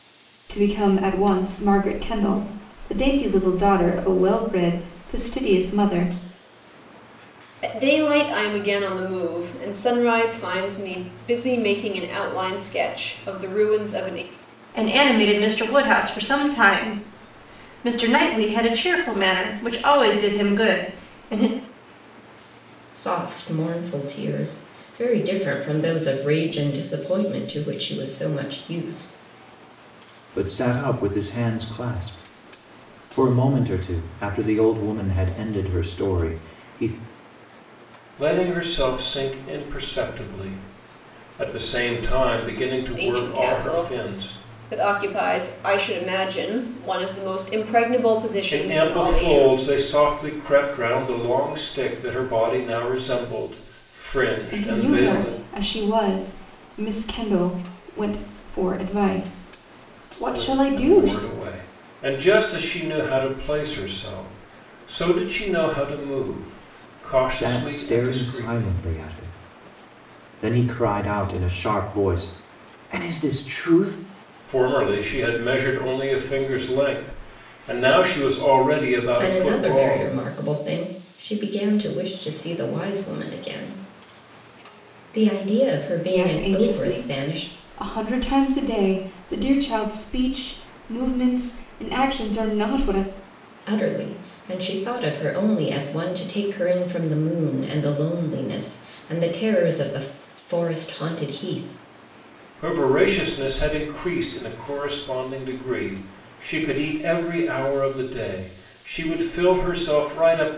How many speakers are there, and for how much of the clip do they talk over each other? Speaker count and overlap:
6, about 7%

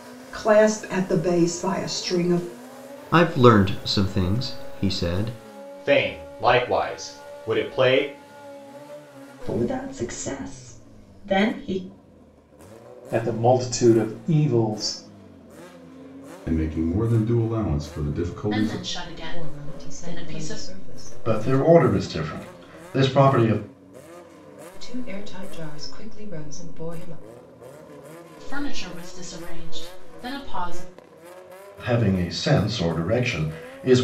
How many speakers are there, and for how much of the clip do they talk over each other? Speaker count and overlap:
9, about 7%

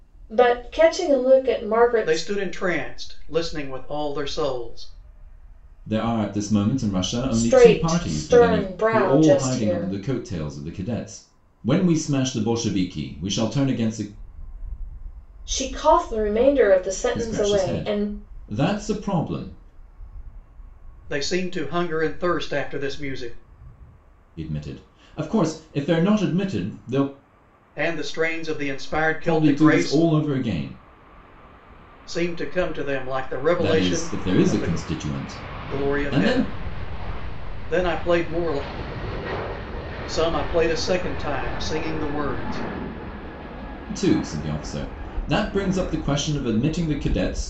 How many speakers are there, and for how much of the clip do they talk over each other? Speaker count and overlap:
3, about 14%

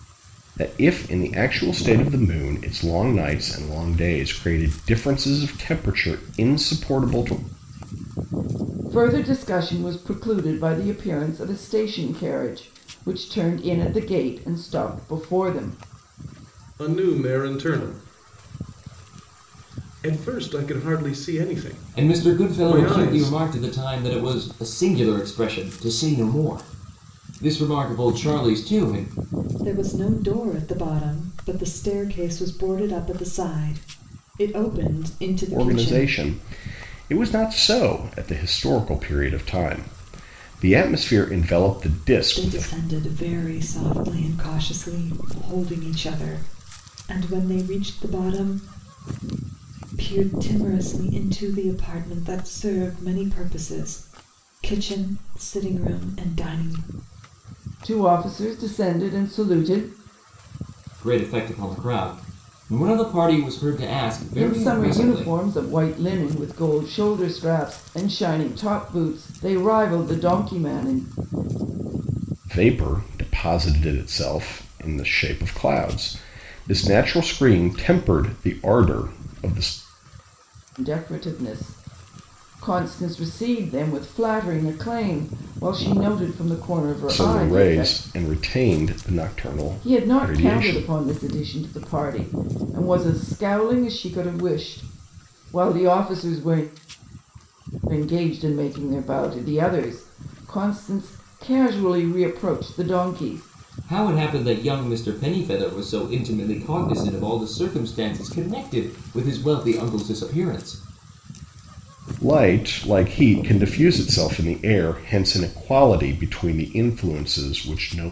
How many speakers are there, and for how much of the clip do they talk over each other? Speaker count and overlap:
5, about 5%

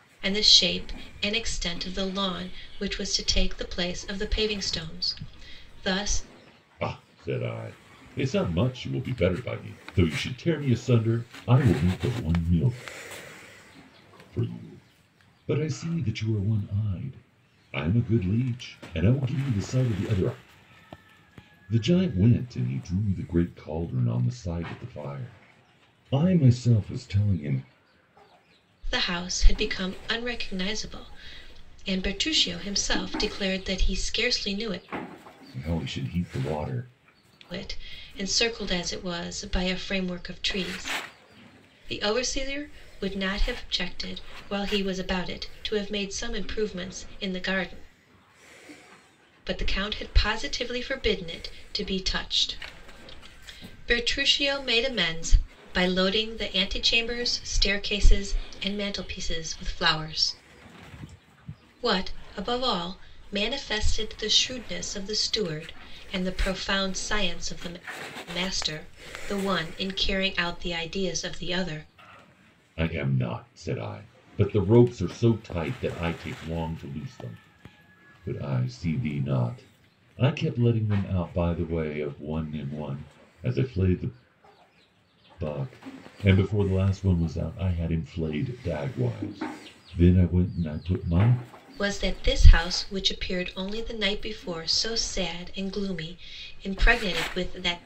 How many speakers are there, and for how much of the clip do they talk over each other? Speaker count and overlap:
2, no overlap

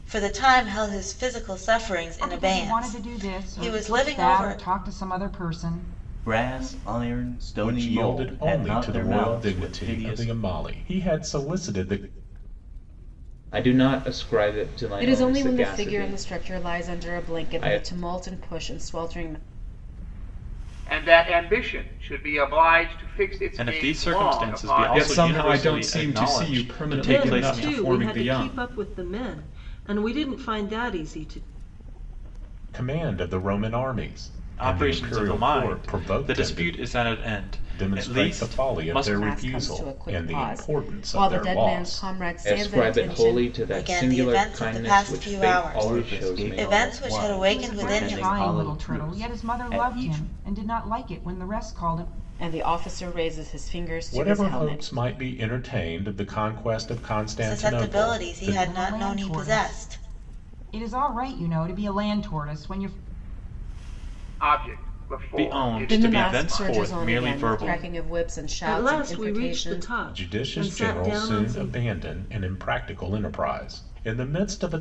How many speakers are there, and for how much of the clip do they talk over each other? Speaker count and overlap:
10, about 50%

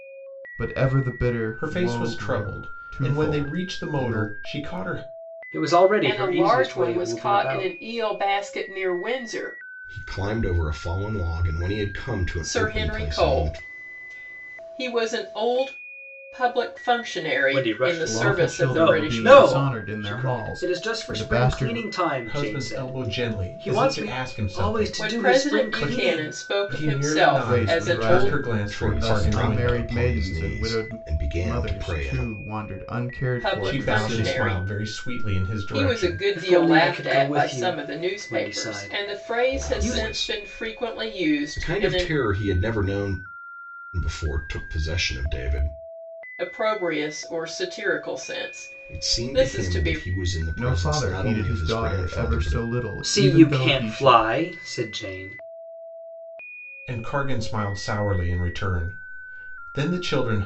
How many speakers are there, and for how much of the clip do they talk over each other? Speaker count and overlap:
5, about 51%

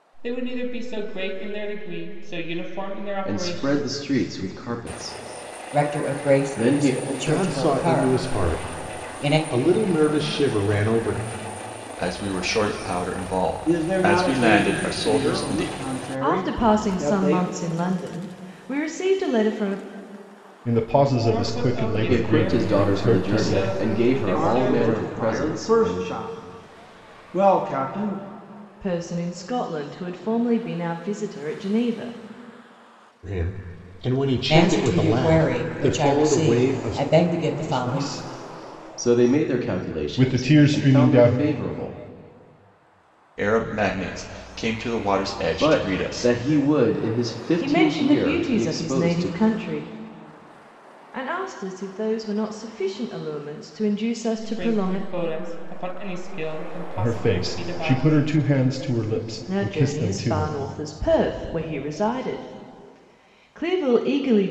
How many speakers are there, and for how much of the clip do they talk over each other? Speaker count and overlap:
8, about 37%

